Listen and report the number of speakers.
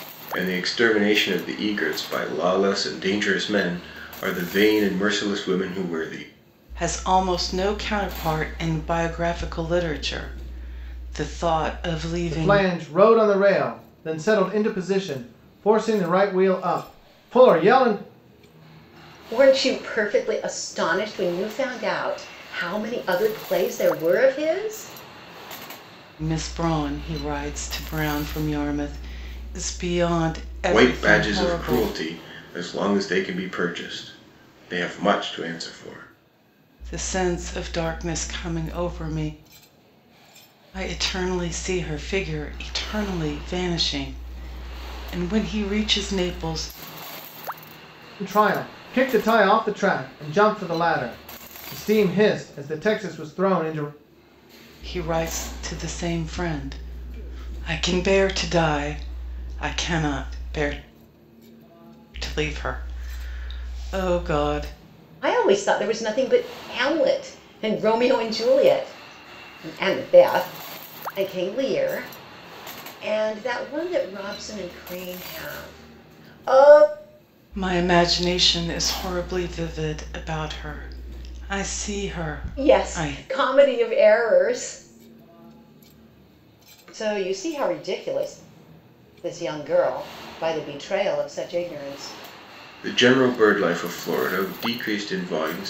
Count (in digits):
4